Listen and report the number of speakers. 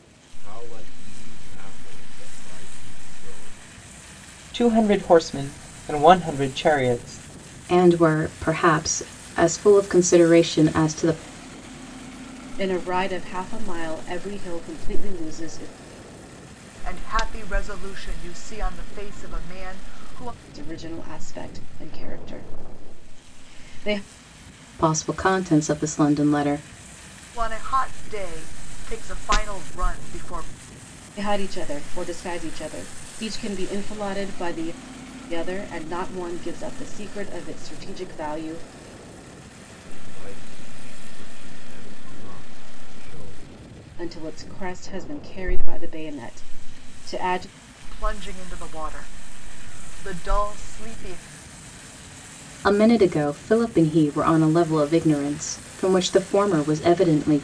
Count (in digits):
5